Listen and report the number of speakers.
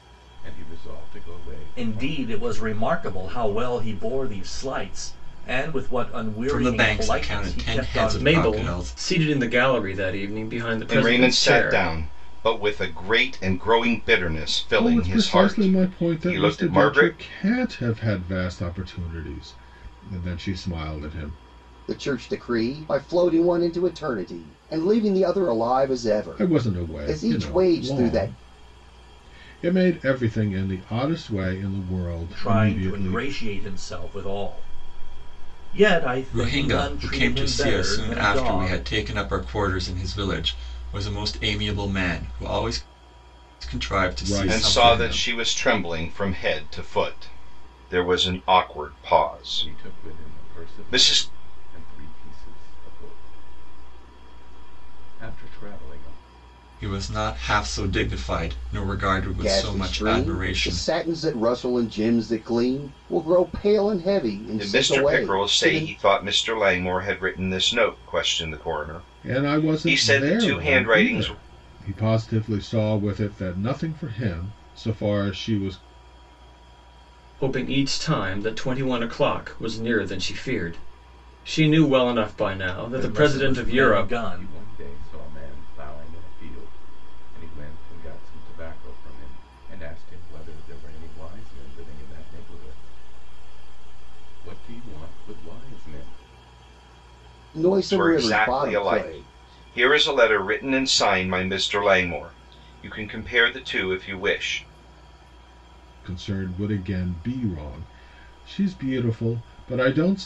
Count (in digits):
7